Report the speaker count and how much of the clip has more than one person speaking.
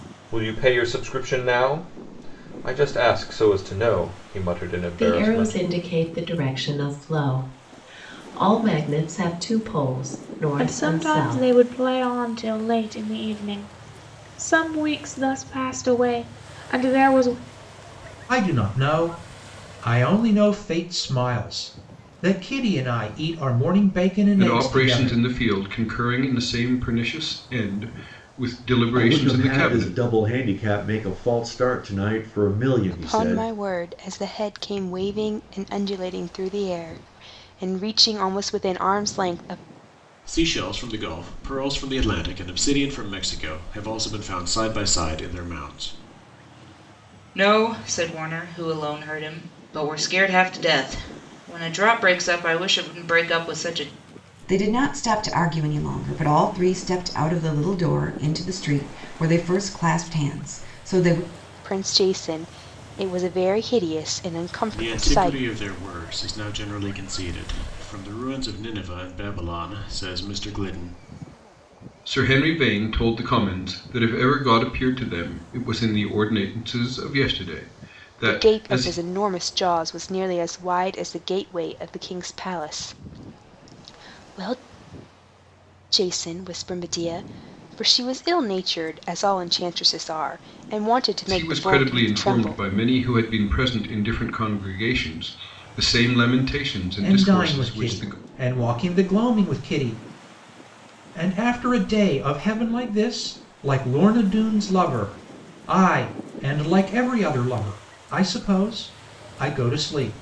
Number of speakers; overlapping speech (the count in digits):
10, about 8%